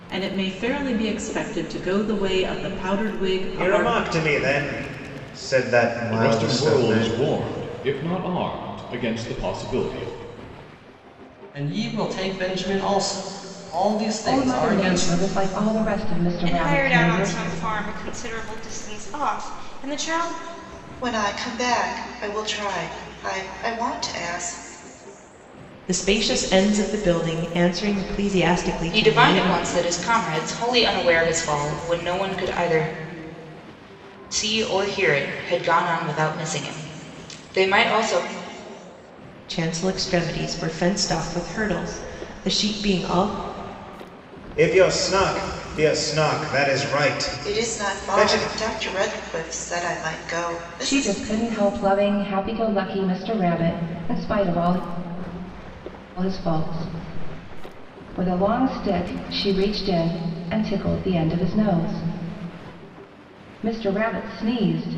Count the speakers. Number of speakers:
9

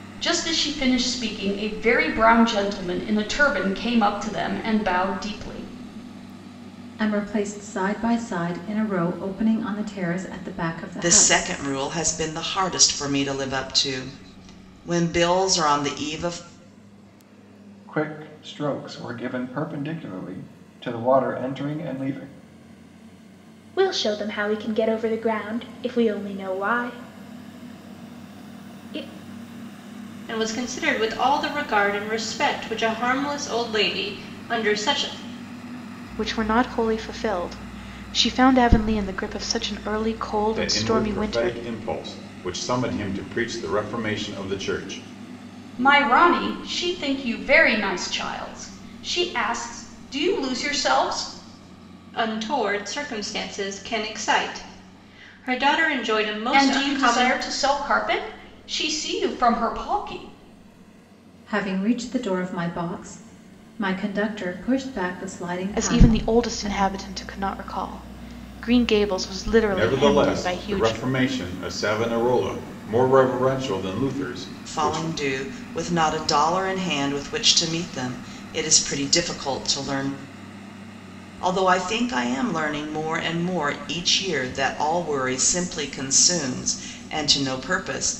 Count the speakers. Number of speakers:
8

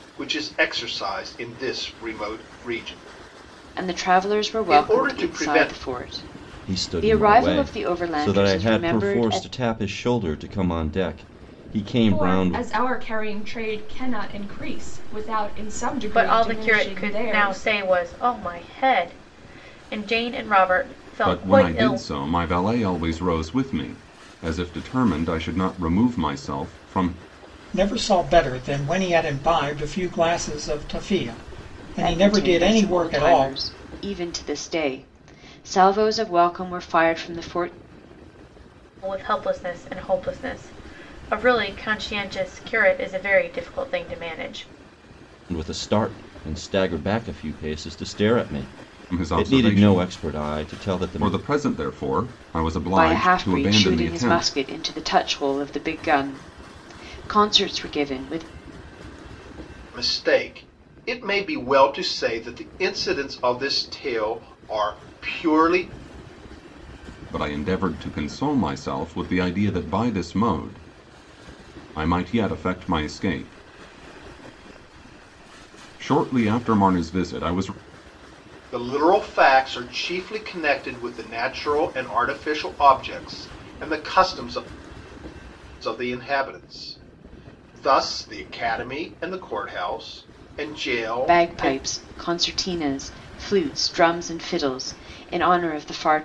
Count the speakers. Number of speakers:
7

